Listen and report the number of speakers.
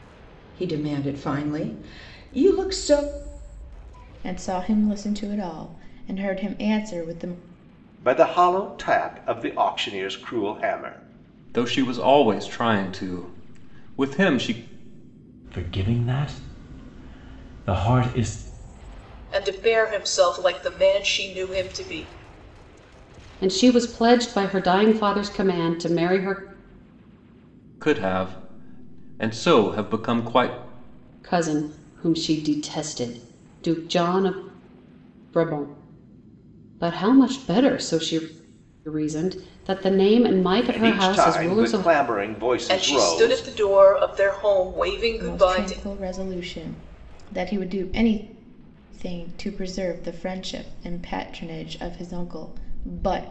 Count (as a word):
seven